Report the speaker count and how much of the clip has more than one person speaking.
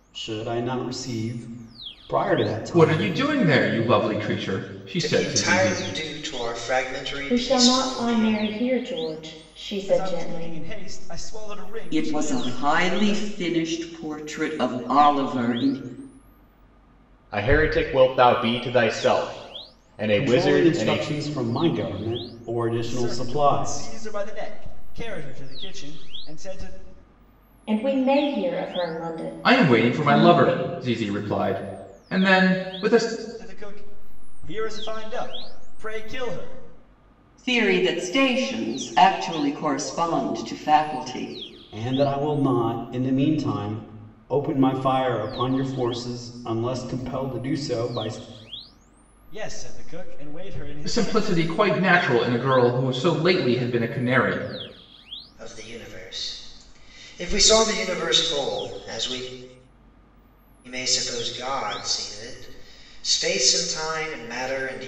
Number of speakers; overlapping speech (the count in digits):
7, about 13%